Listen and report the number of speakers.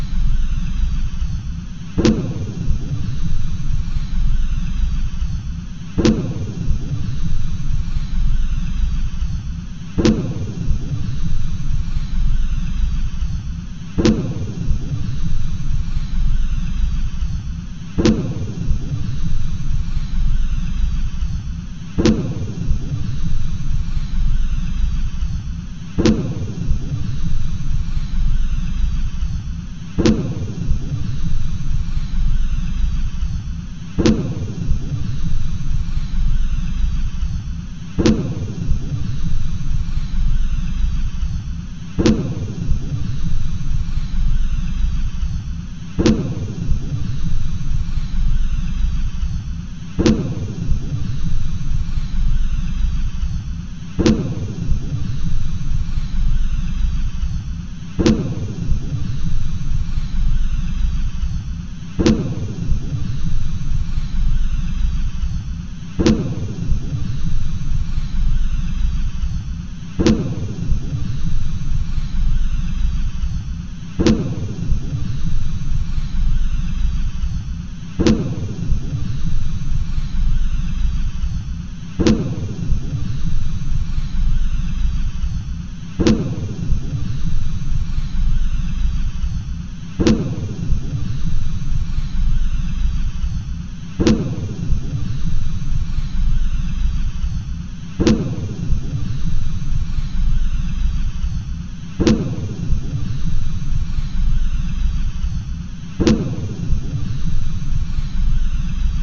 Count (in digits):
0